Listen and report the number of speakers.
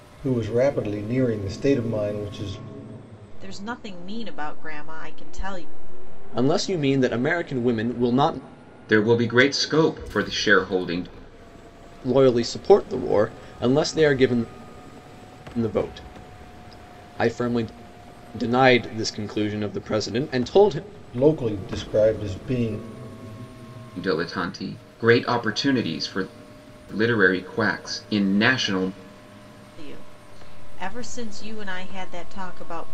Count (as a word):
four